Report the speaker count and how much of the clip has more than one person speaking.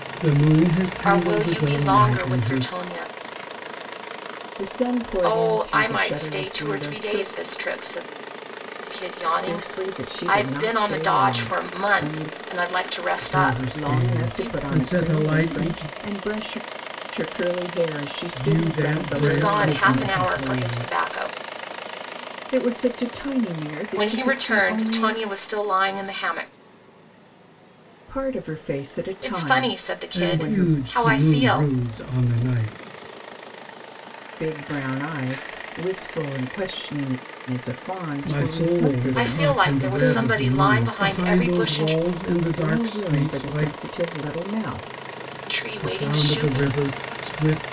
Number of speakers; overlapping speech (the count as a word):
three, about 46%